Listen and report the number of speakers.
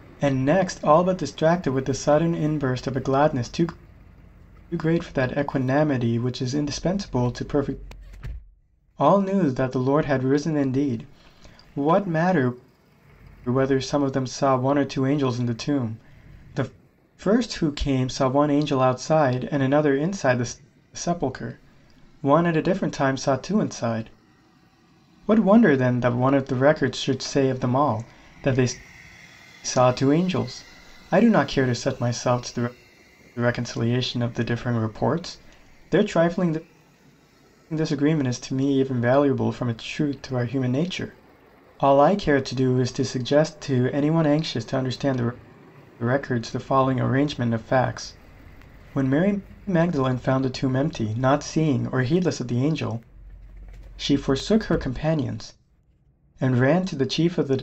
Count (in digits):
1